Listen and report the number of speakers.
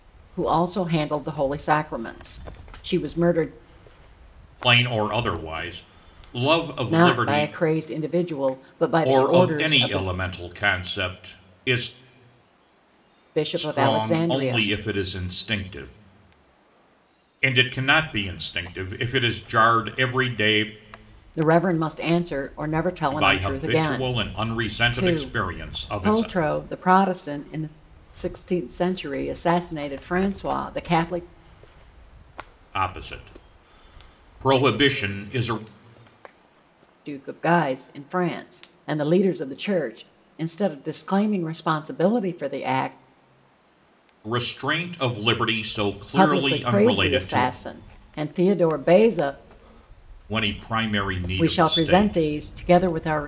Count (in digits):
2